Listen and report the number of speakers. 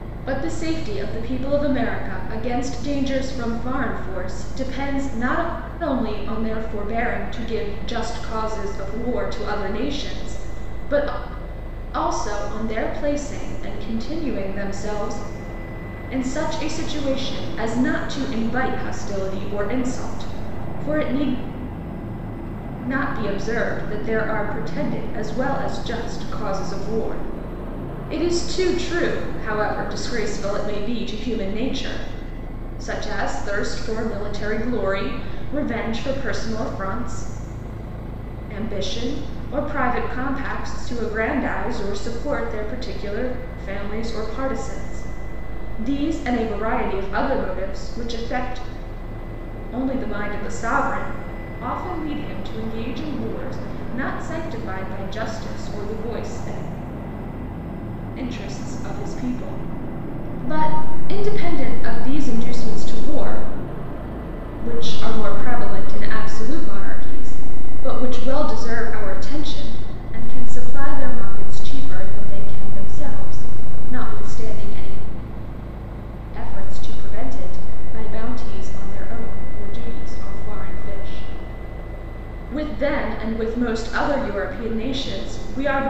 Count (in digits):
1